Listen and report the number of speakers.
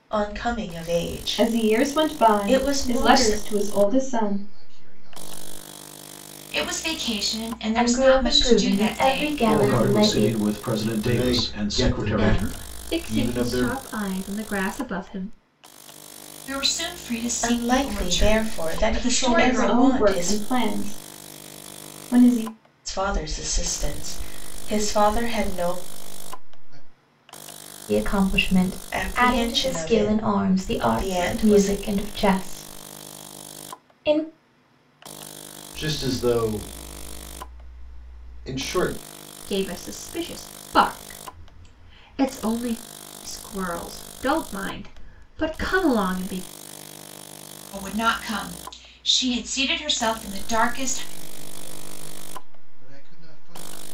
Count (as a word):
eight